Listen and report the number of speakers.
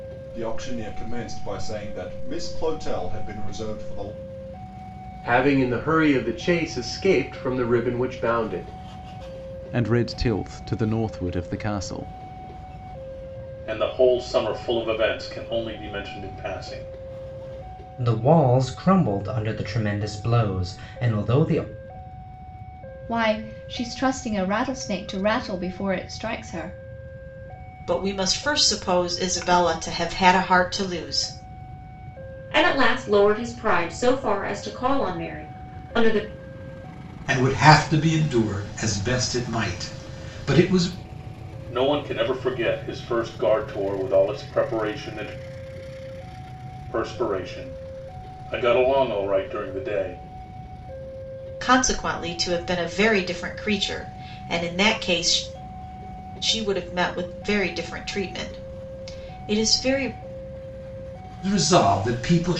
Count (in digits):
9